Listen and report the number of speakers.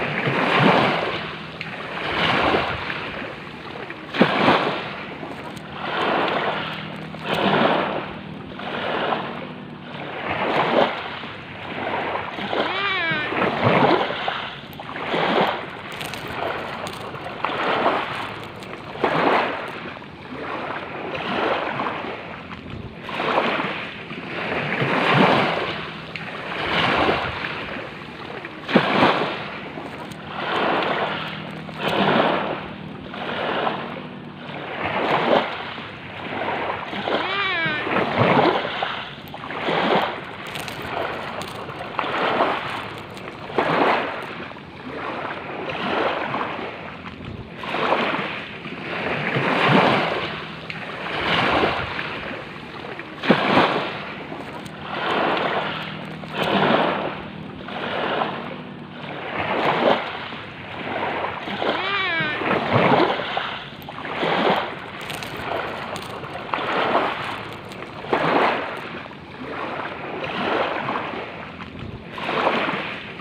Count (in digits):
0